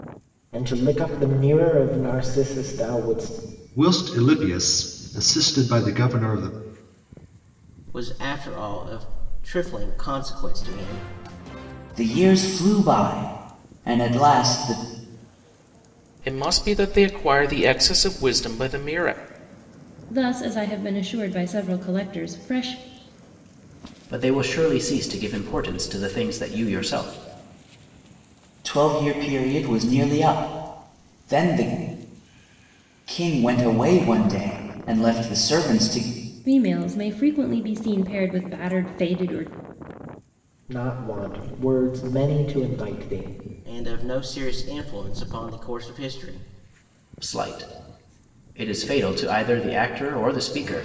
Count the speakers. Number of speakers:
seven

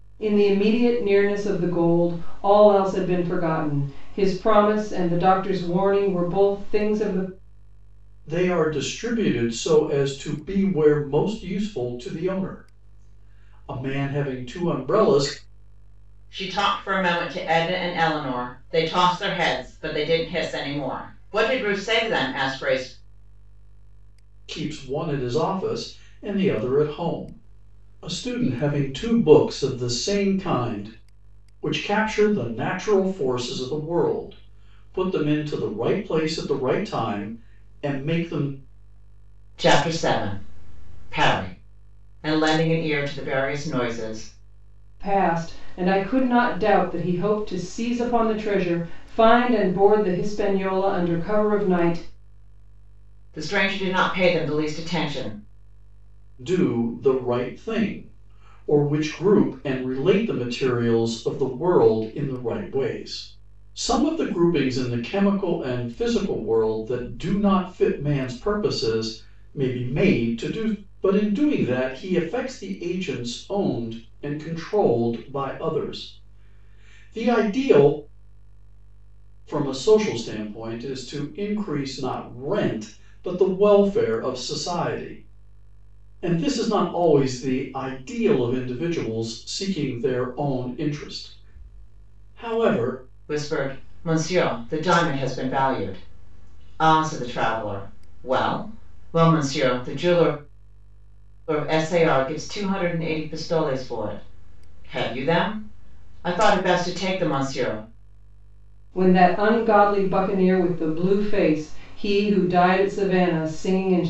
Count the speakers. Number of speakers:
three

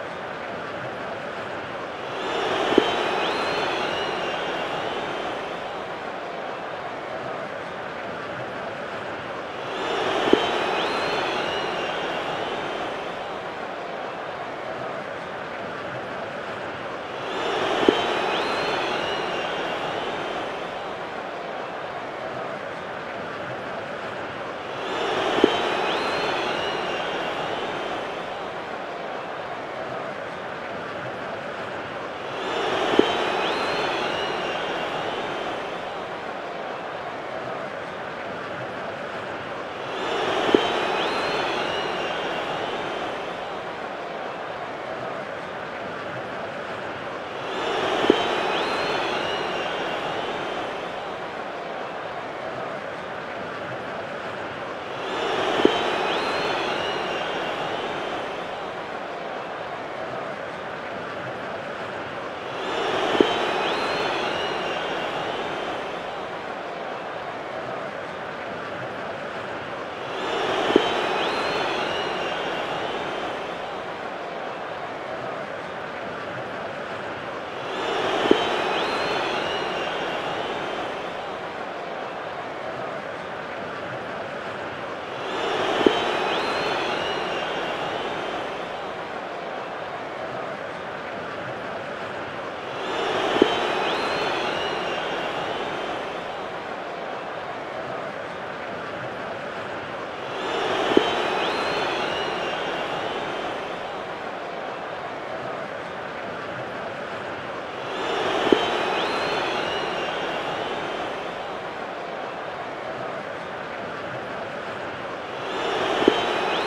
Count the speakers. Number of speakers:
zero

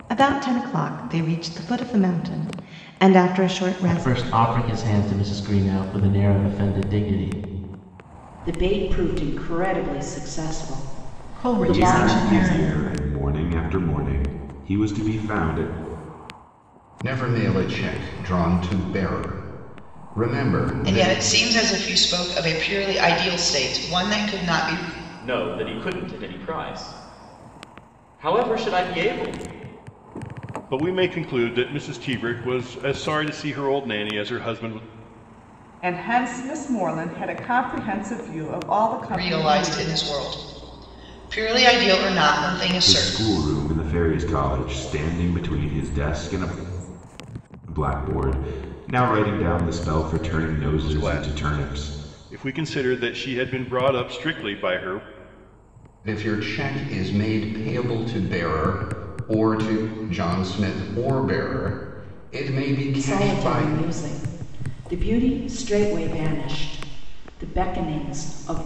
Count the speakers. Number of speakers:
ten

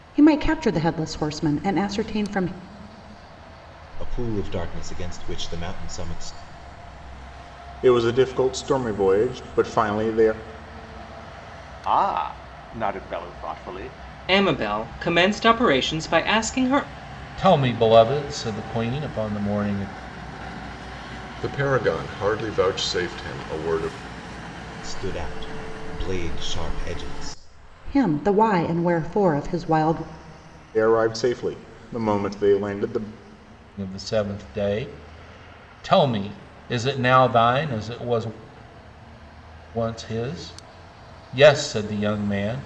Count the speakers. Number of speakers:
seven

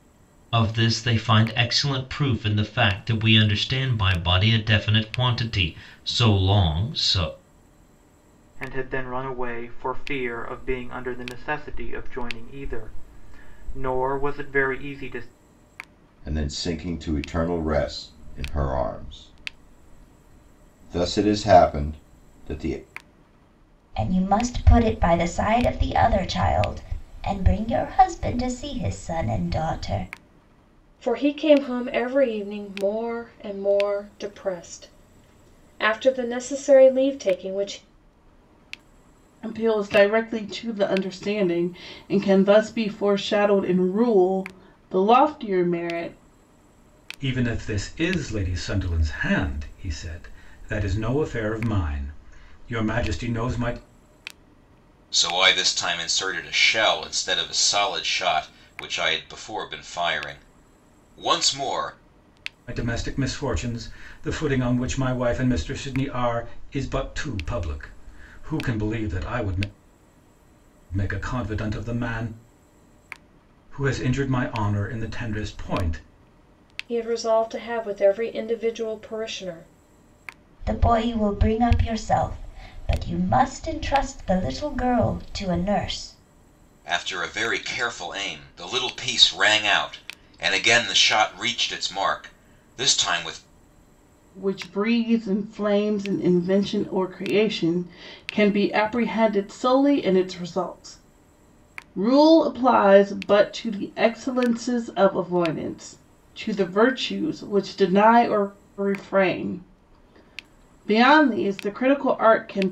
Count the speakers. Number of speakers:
eight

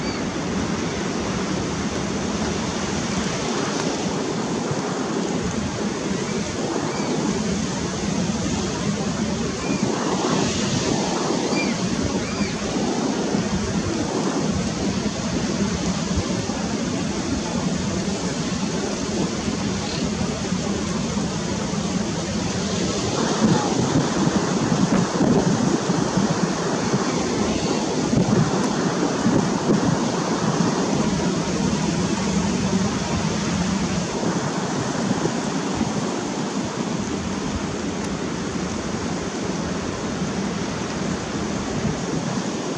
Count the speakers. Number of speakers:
zero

